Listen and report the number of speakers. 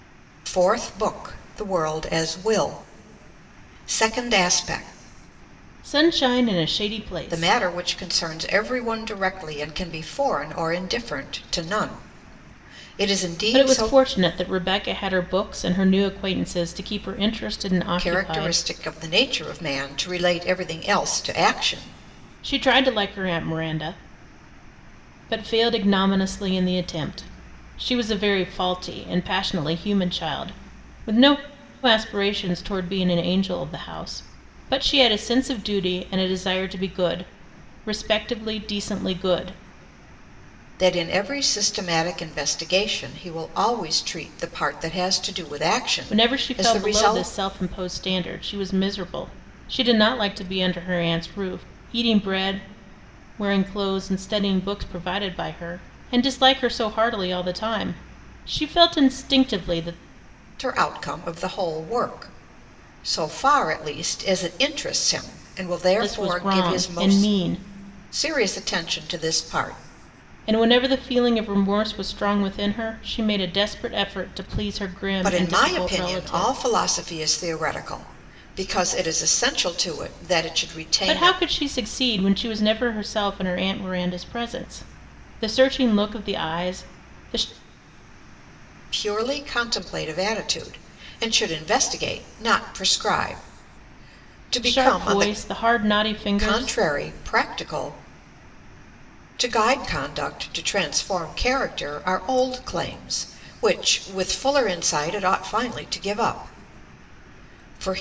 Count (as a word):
two